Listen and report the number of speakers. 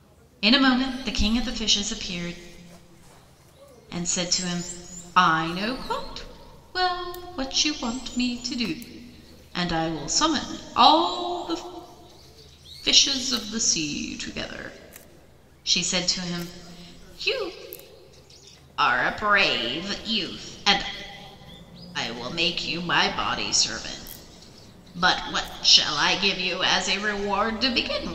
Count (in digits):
1